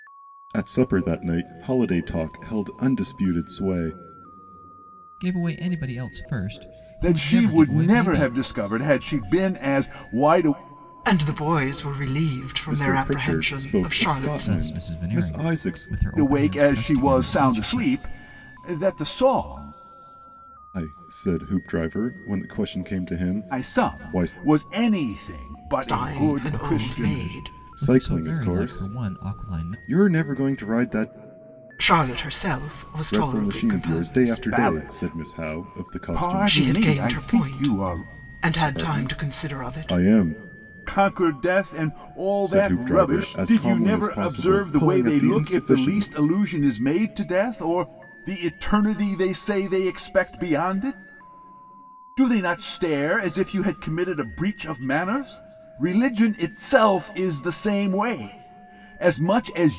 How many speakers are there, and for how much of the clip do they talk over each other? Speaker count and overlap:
4, about 35%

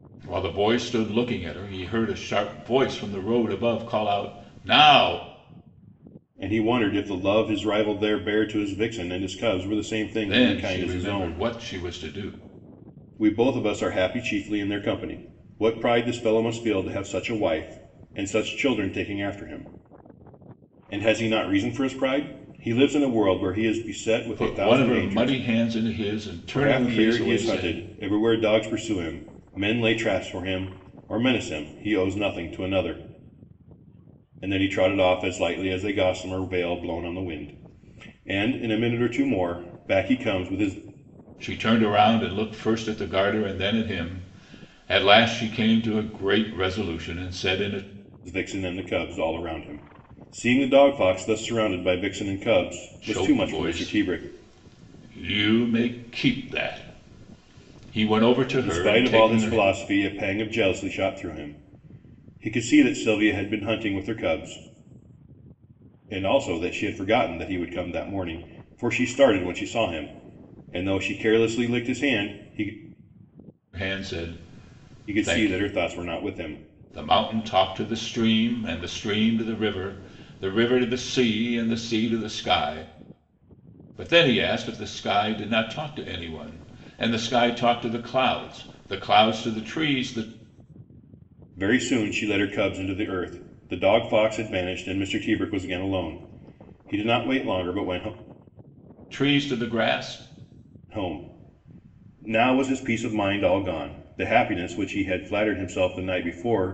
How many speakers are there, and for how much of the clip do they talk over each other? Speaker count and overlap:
2, about 6%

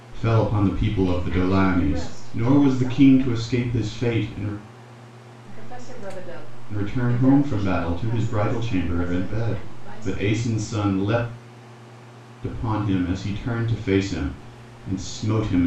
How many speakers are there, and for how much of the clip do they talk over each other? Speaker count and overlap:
2, about 37%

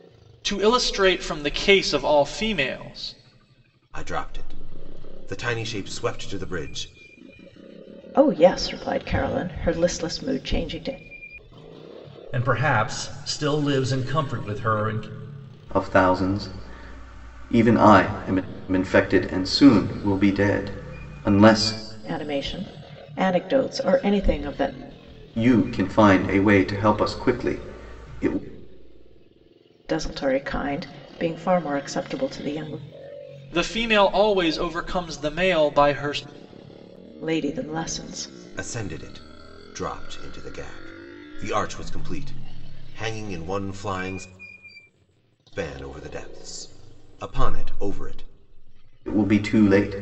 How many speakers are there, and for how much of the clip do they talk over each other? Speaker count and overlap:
5, no overlap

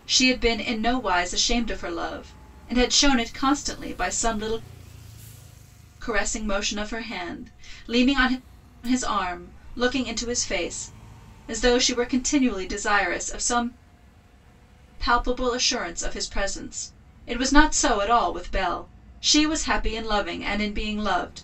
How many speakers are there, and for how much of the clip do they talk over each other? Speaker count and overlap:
1, no overlap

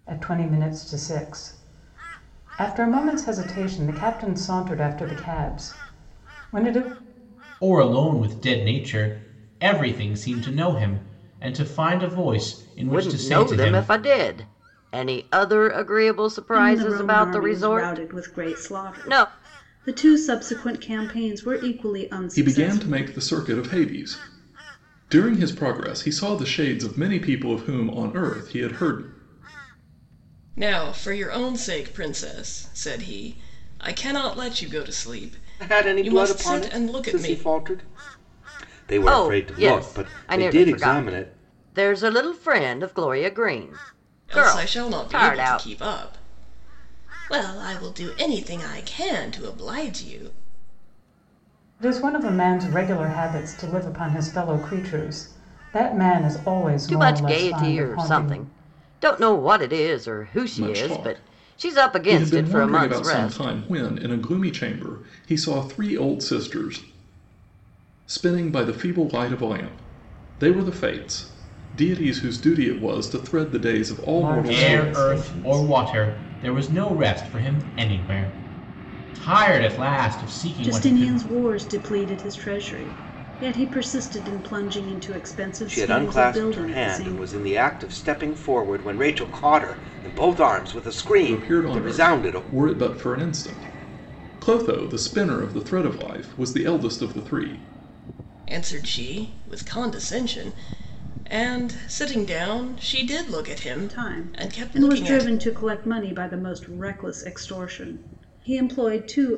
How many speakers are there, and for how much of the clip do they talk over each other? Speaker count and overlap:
7, about 19%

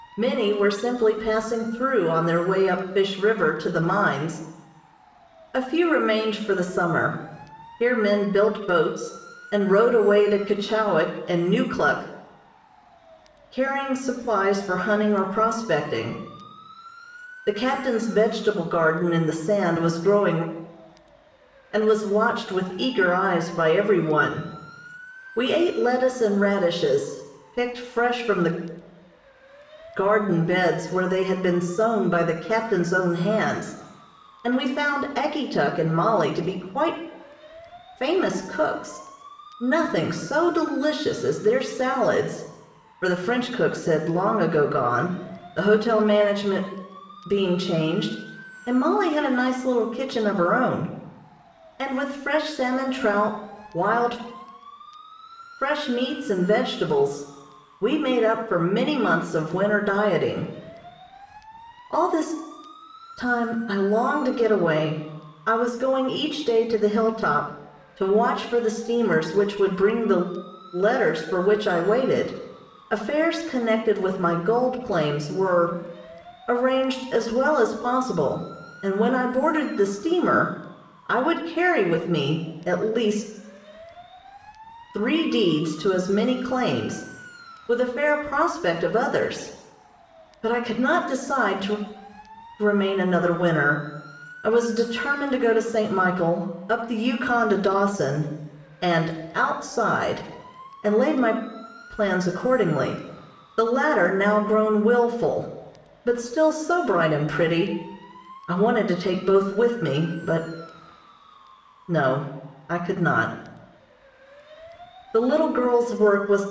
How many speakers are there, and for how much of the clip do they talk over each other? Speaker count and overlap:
1, no overlap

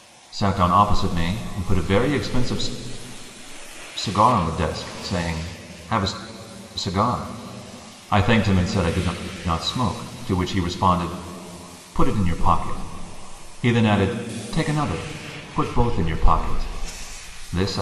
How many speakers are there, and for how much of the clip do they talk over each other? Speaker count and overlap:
1, no overlap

